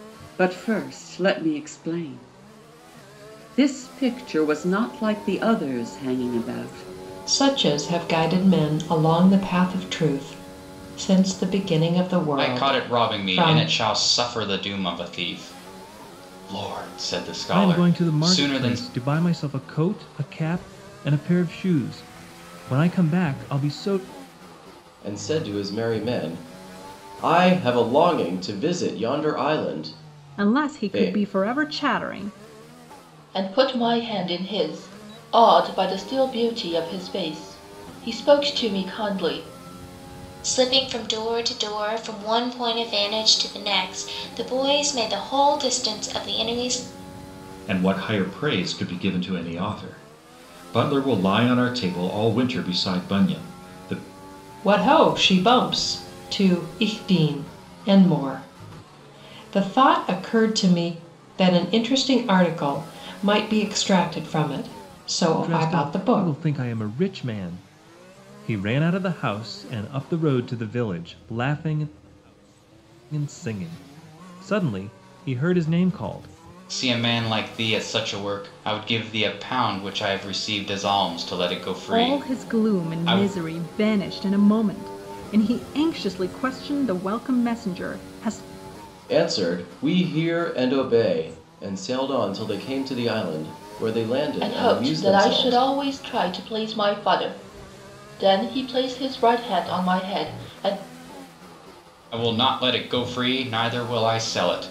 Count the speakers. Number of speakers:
nine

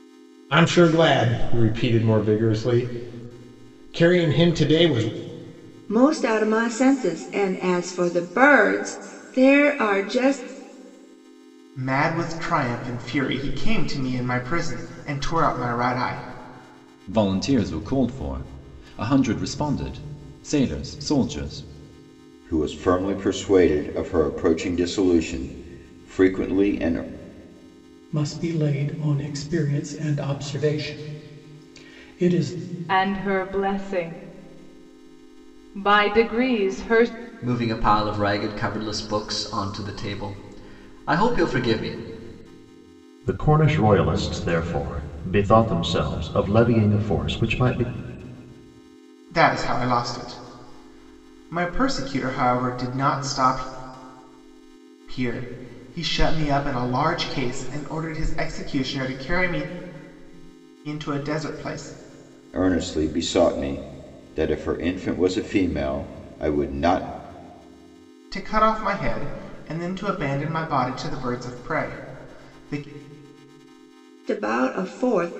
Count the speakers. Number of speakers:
nine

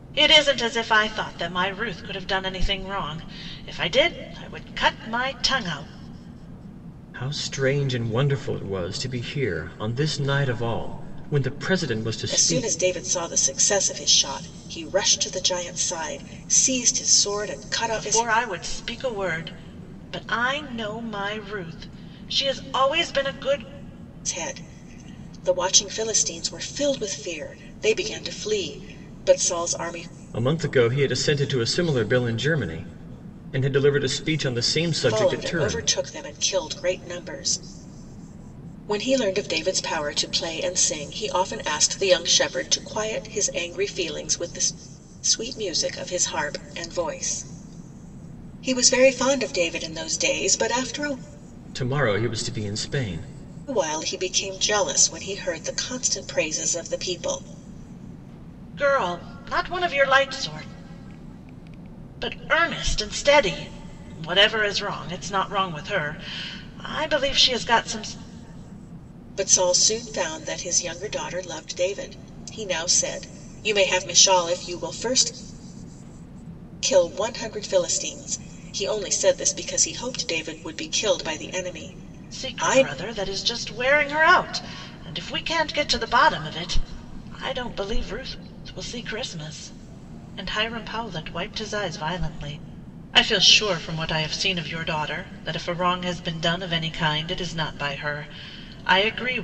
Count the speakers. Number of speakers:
three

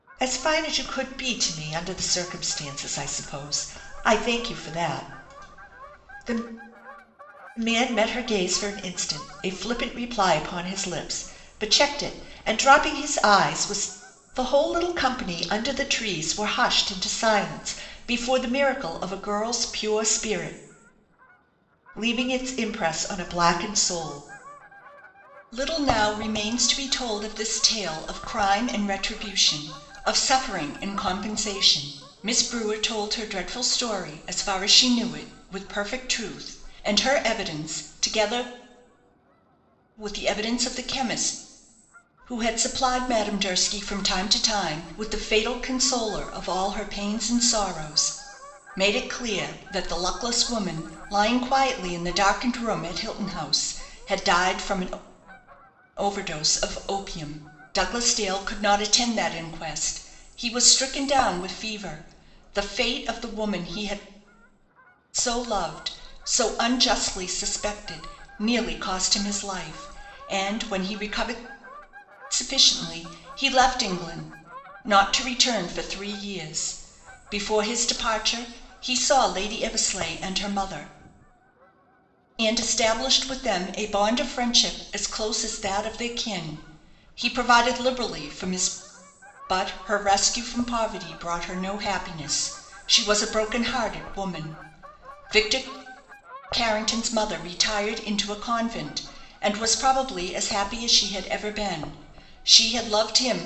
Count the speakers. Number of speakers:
one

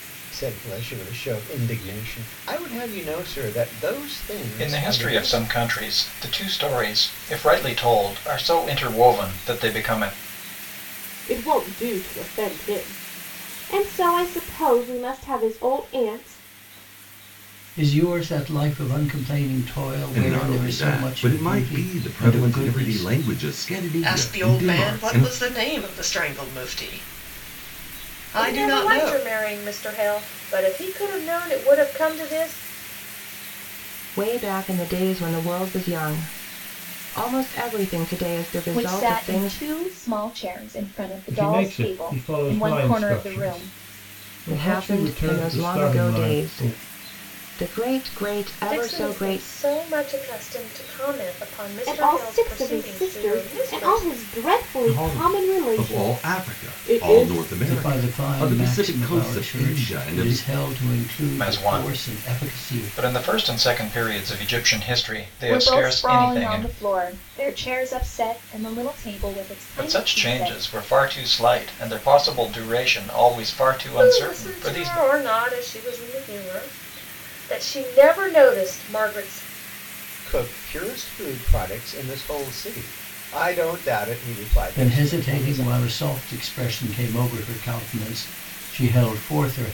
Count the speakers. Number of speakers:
ten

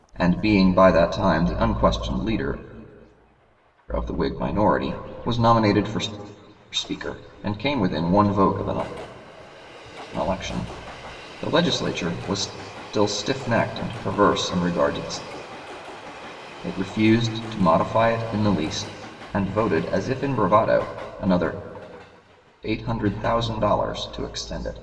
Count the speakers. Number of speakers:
one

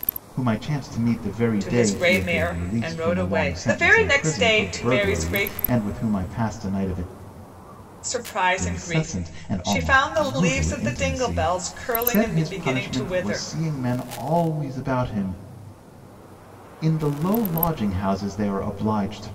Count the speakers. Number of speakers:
two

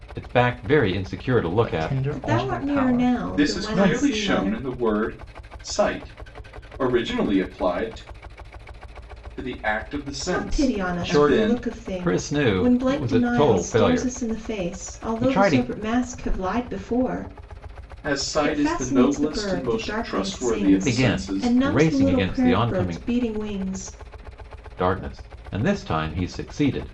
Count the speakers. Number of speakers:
four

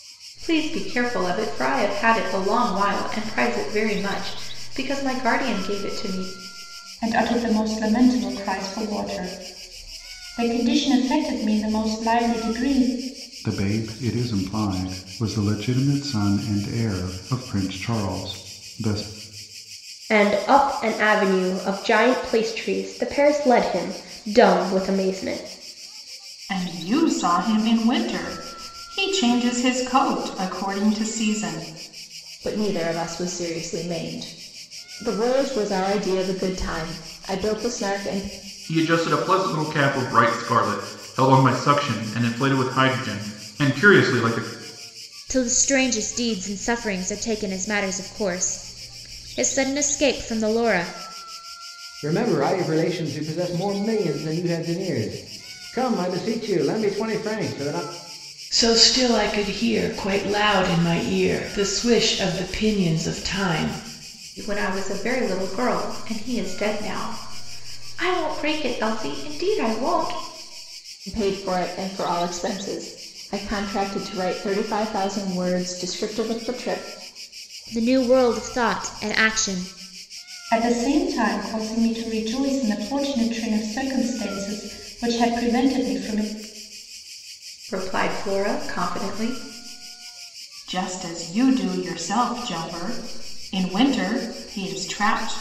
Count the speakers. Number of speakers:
ten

